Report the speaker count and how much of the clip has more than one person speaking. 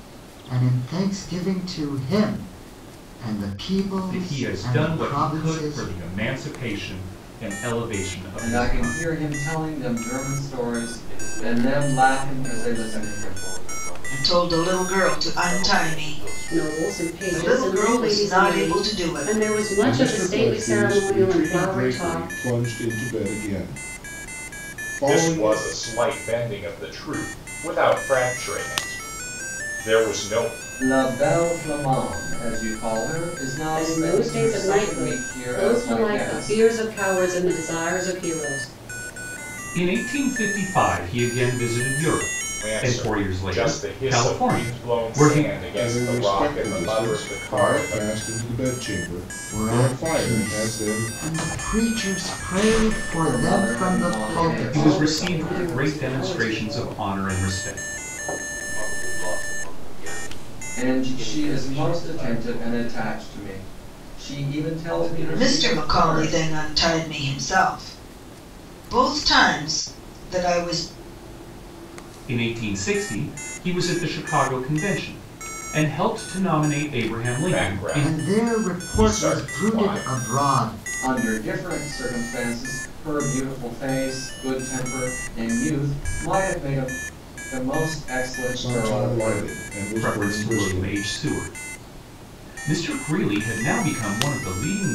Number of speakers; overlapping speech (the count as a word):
eight, about 39%